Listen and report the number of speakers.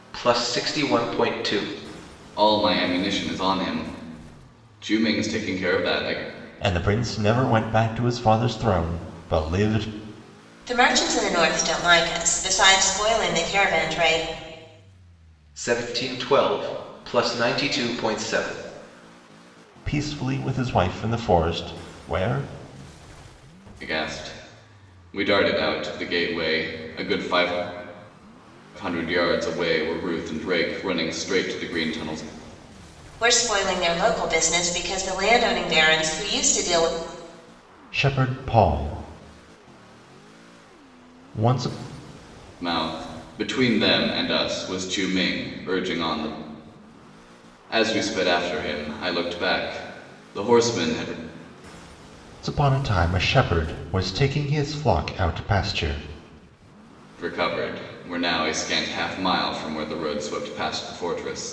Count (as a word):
four